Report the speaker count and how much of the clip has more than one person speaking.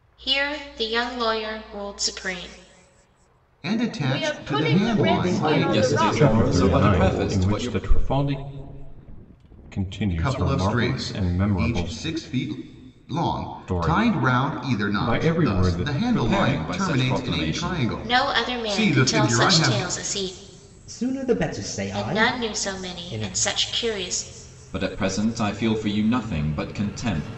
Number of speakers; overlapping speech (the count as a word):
seven, about 48%